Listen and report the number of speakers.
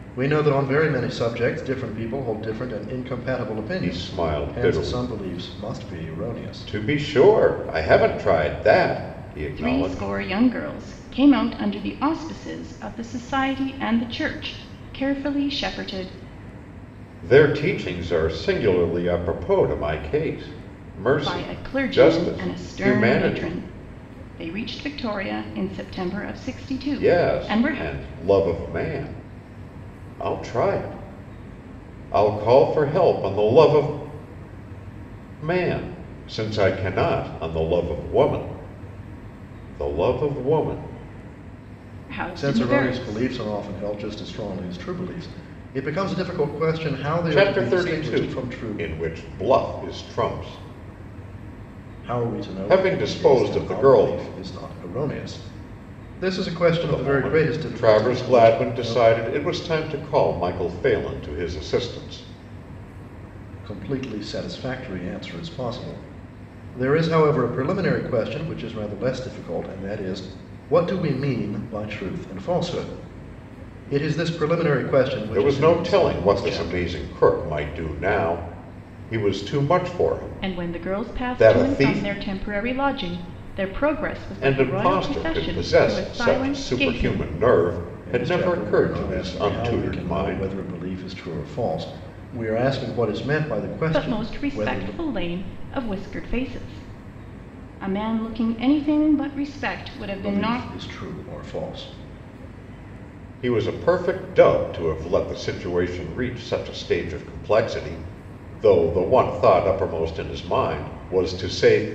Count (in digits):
3